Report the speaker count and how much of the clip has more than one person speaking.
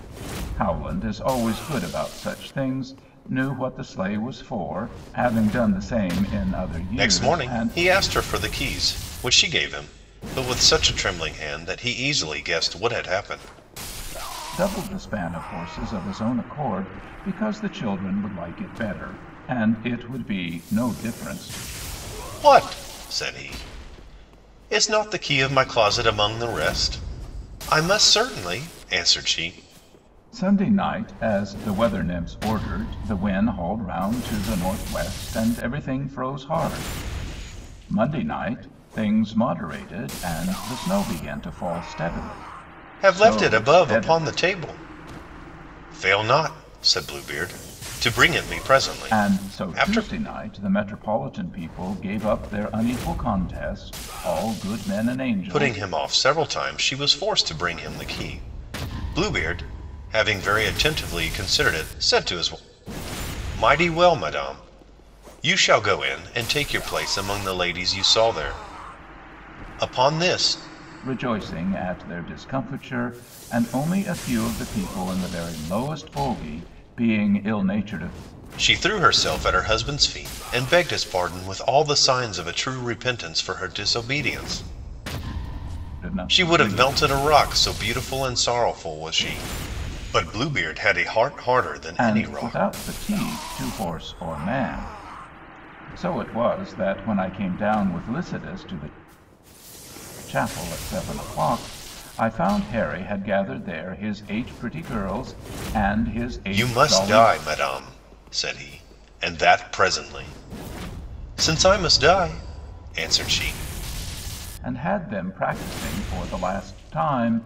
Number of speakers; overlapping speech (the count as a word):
two, about 5%